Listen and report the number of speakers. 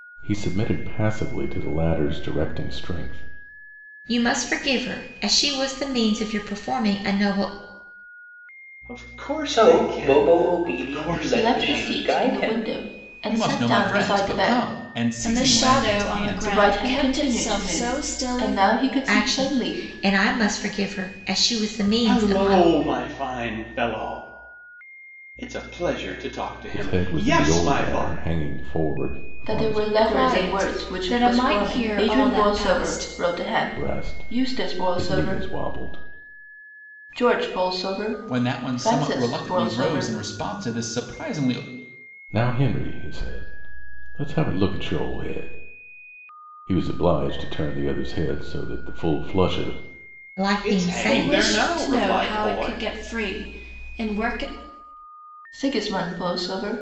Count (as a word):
seven